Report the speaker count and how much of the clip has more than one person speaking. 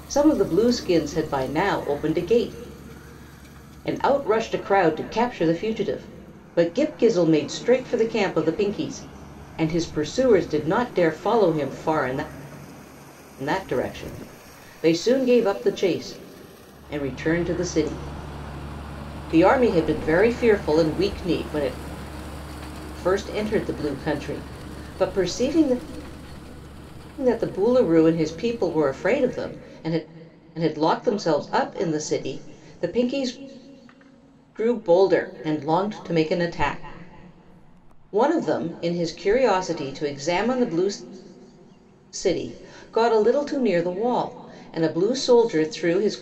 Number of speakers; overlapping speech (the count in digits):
1, no overlap